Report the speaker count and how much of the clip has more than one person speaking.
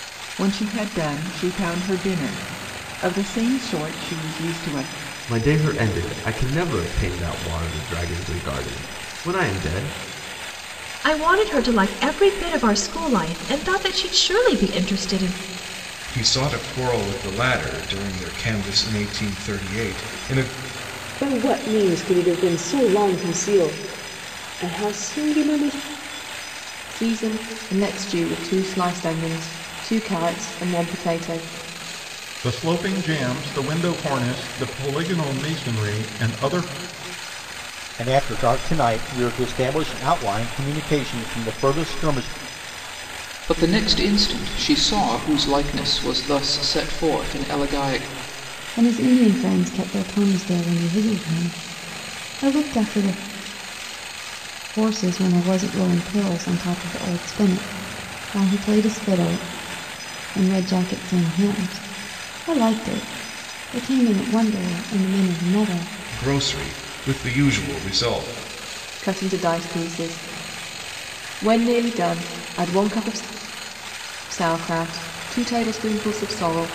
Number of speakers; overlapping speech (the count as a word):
ten, no overlap